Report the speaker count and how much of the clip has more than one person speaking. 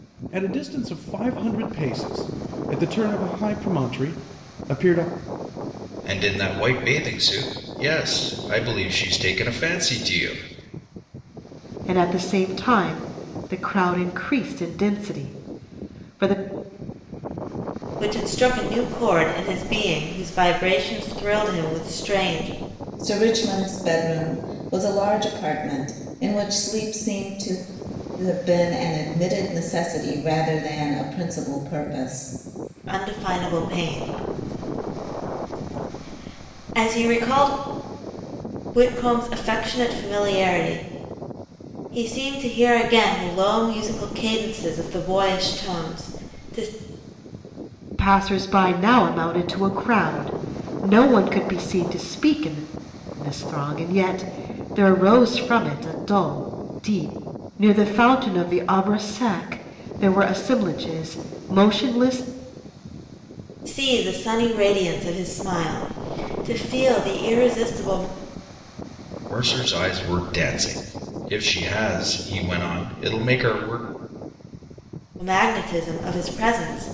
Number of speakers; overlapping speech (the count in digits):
5, no overlap